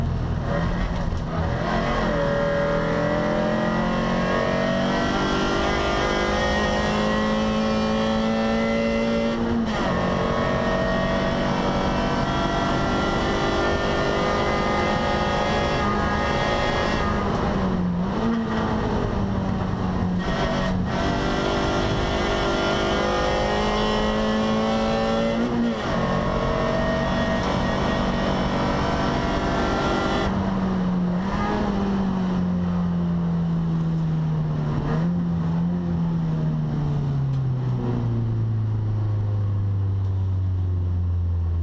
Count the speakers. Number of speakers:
zero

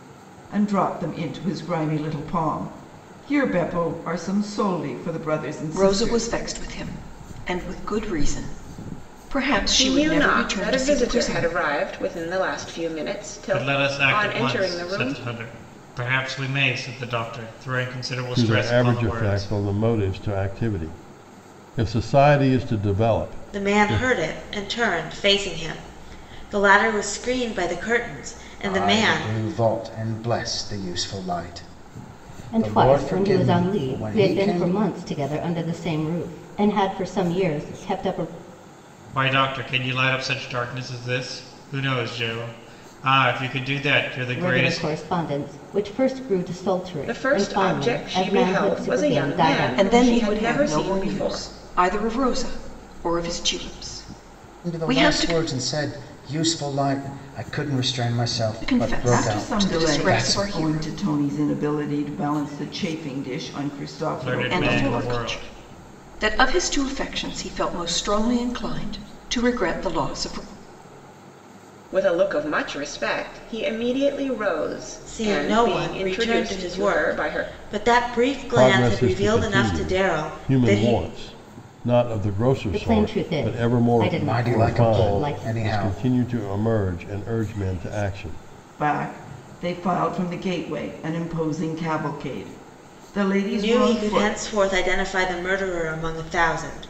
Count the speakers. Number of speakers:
eight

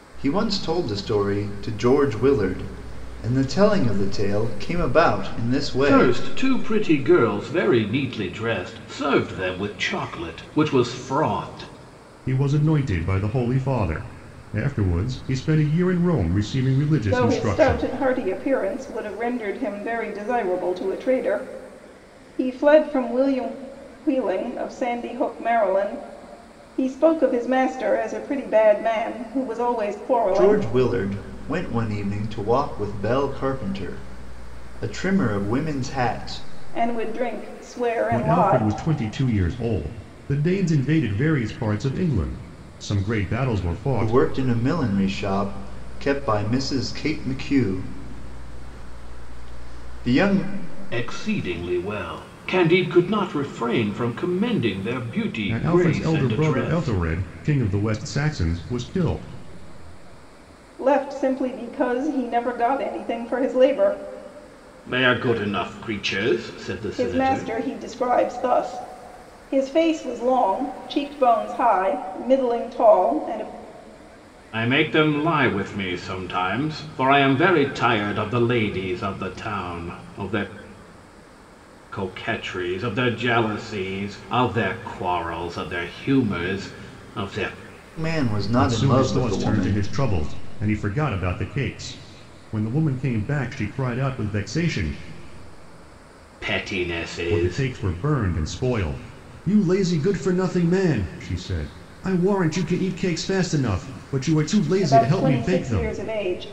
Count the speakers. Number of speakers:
four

